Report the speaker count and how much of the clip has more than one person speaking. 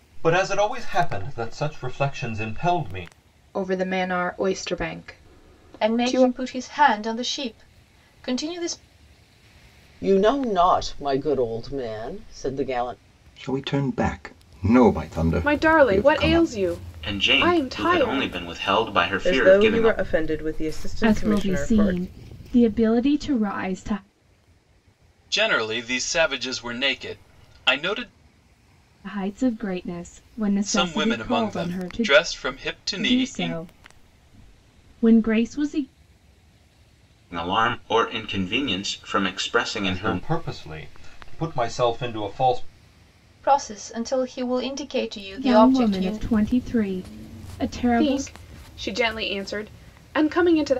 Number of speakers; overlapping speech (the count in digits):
10, about 17%